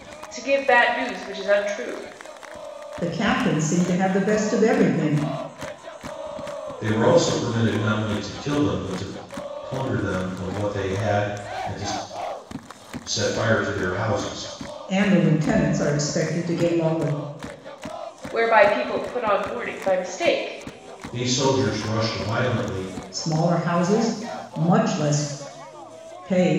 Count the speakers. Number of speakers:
three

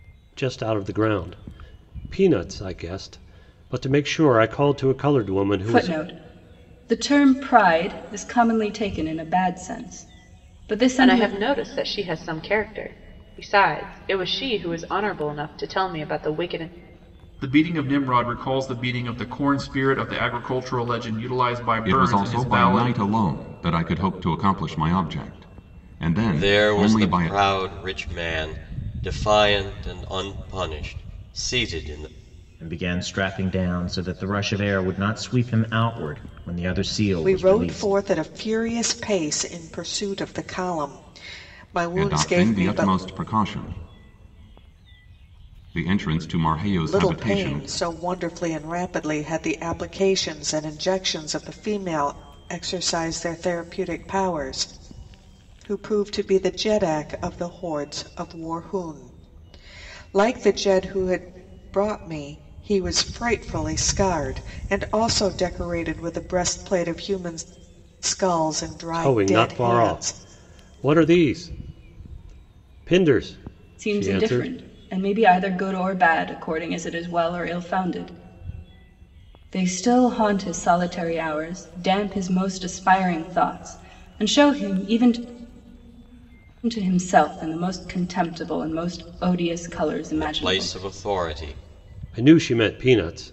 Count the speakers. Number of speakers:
eight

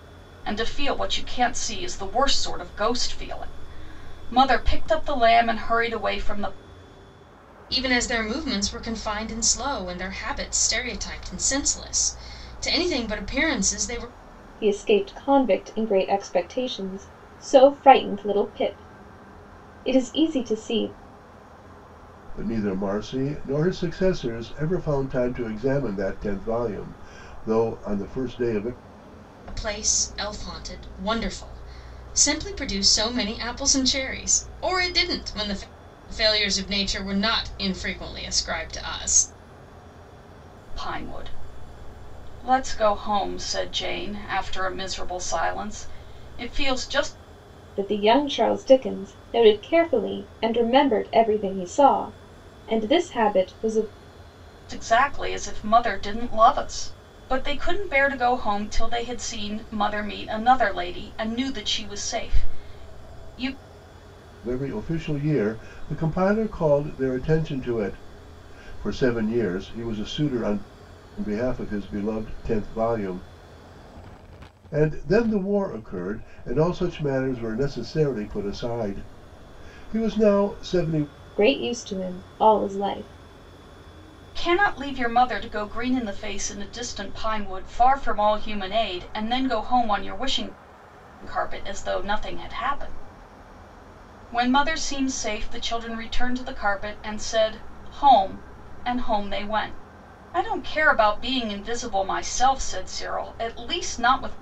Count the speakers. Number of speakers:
four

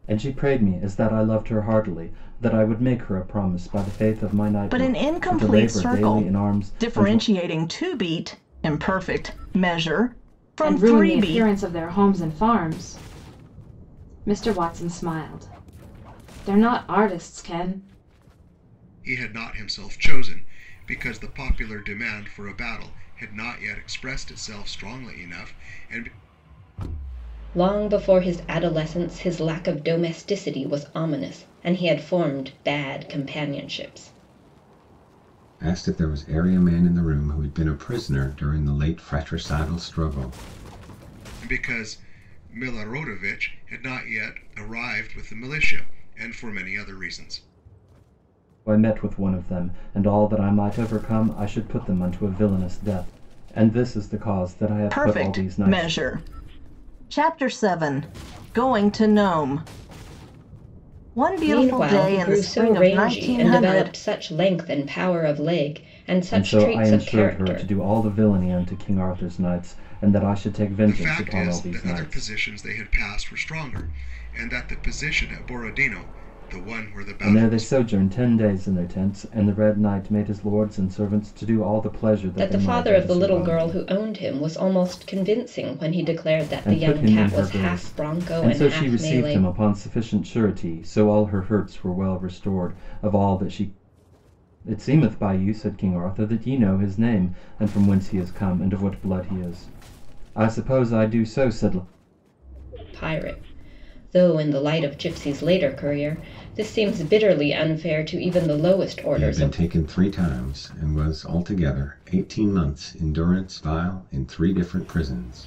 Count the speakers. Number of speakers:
six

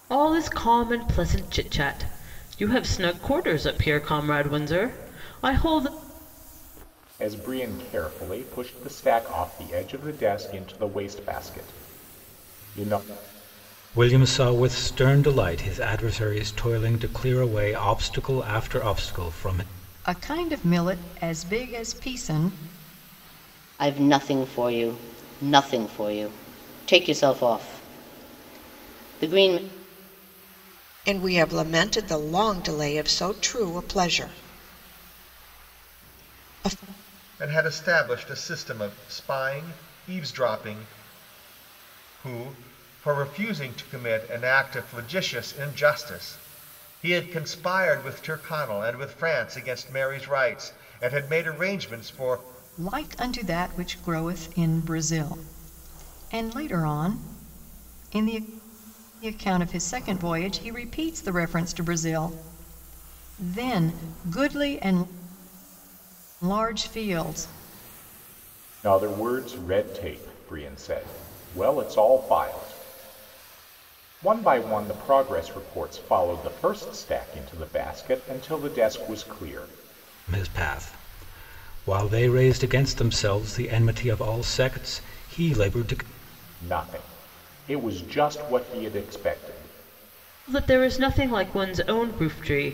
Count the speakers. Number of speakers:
seven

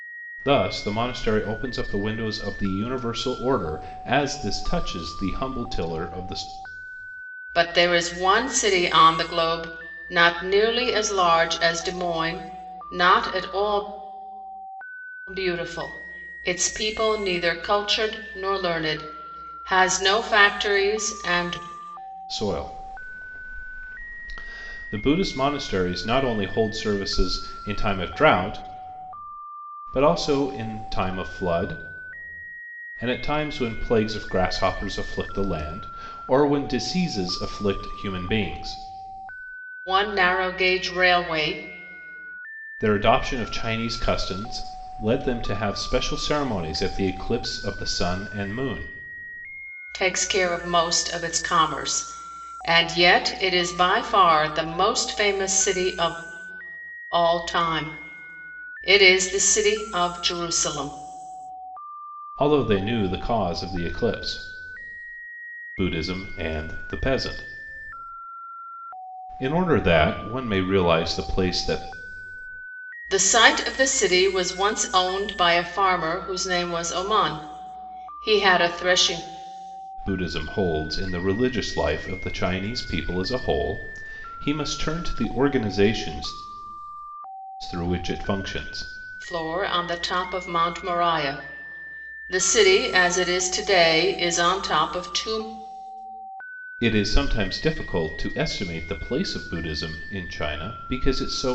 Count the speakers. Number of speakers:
two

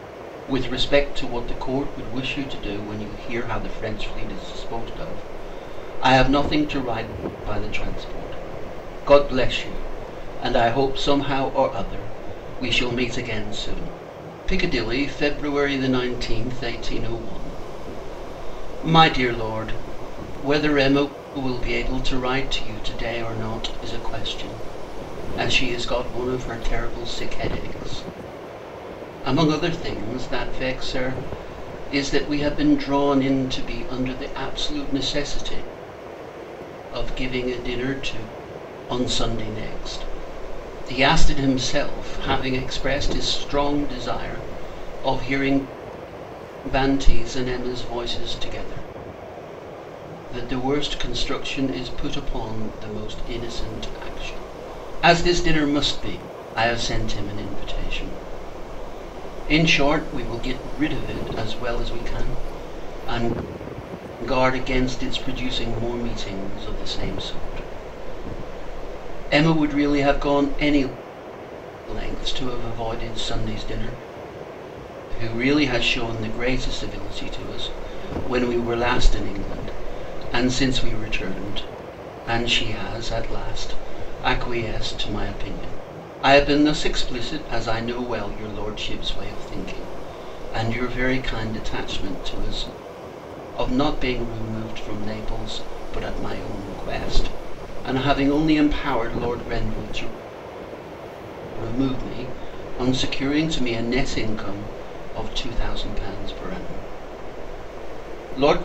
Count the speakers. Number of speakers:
one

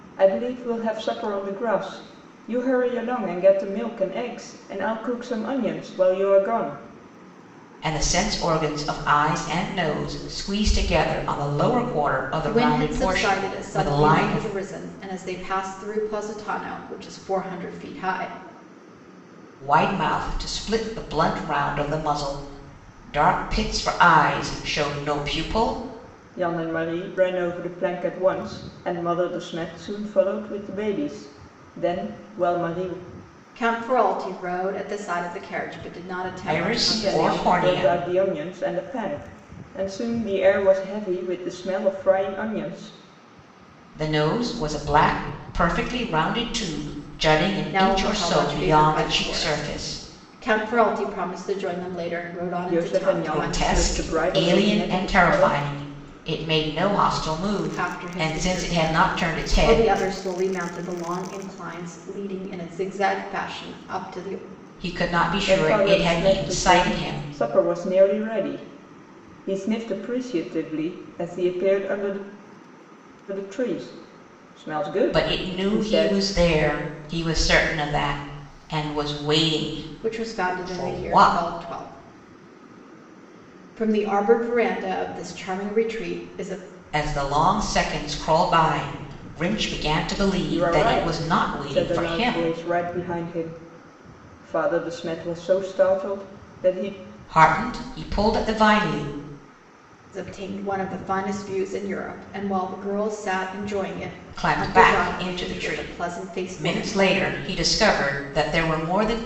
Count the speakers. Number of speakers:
three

